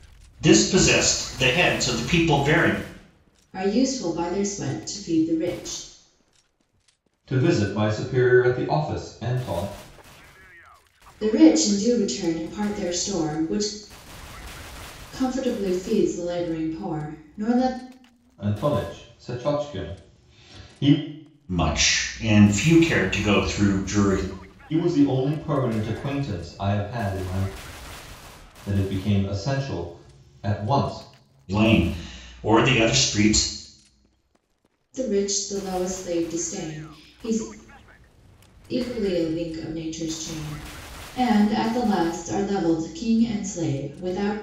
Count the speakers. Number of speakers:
3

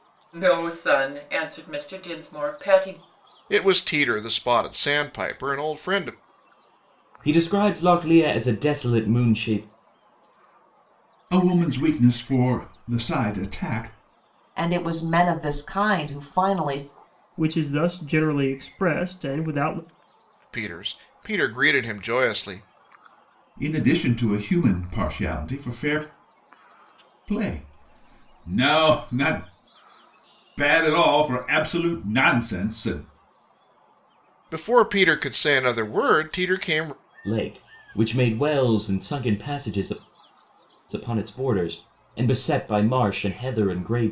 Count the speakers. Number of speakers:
6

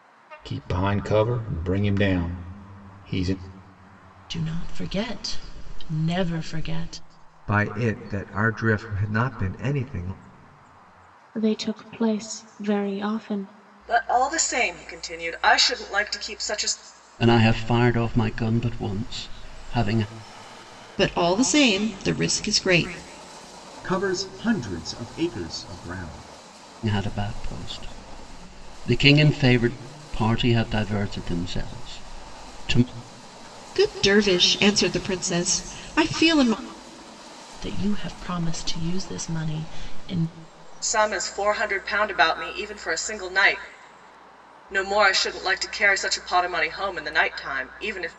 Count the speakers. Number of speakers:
8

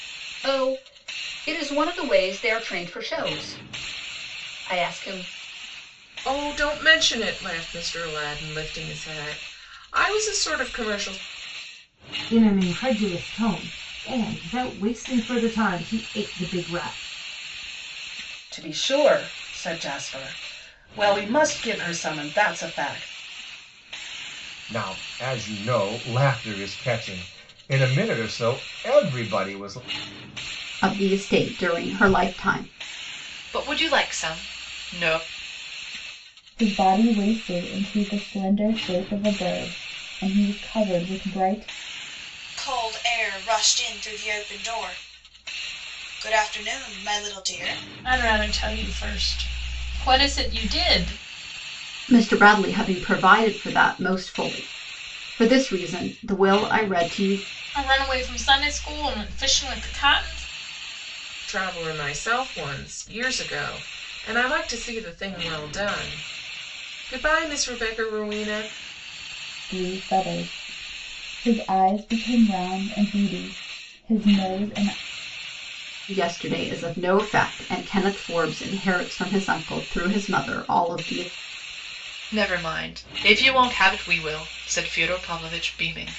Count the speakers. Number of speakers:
10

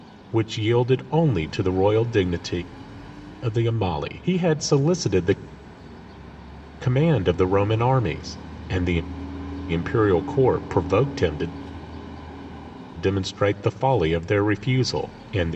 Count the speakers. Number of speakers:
1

